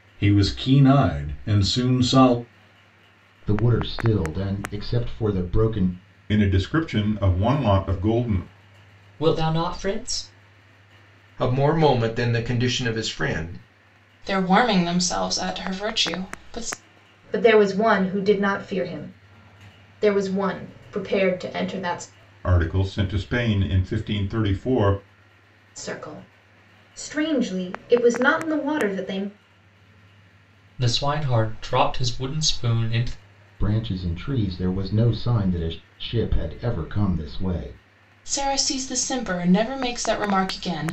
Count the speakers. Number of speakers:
7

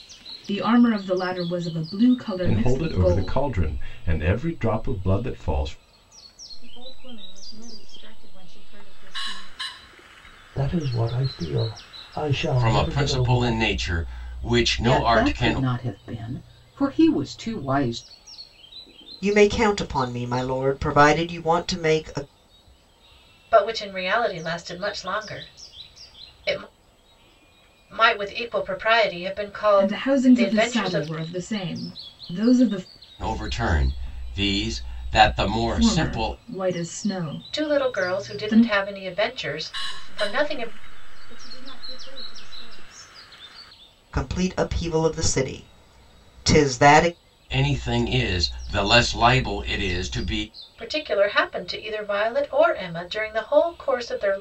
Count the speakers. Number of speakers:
8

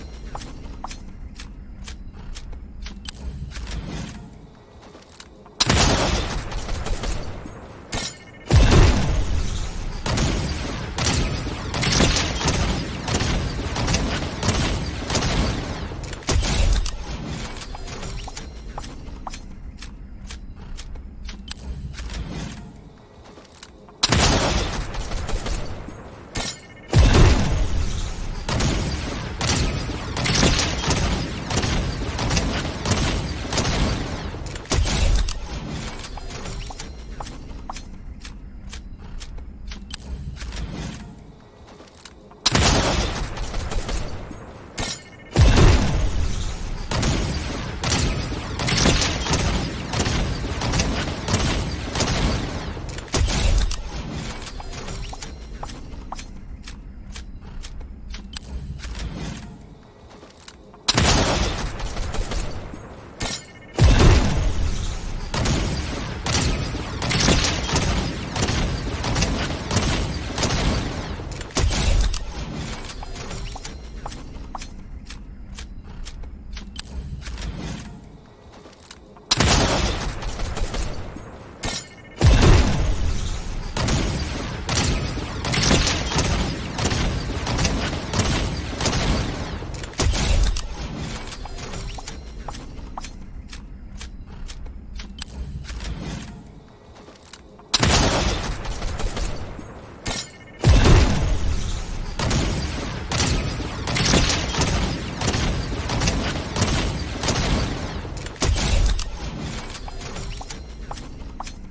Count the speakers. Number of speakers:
0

